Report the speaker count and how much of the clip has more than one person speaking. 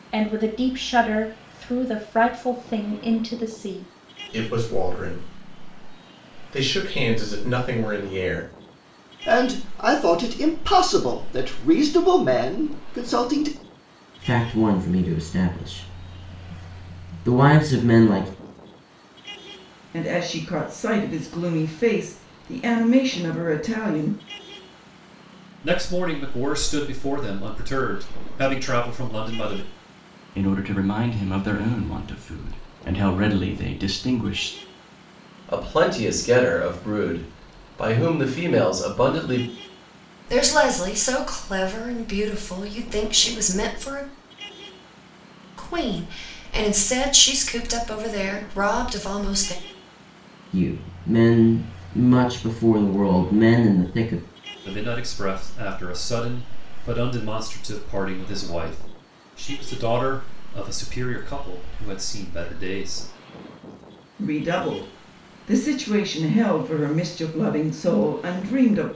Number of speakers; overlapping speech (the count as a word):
nine, no overlap